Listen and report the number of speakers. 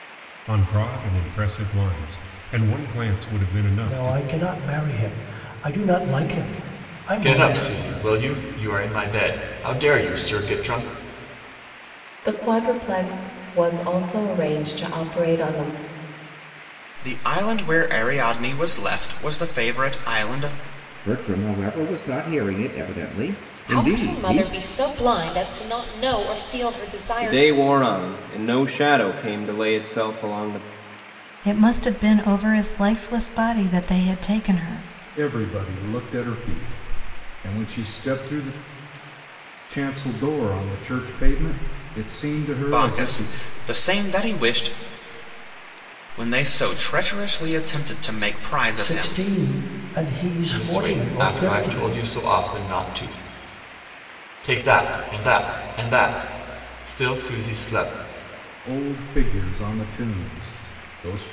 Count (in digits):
10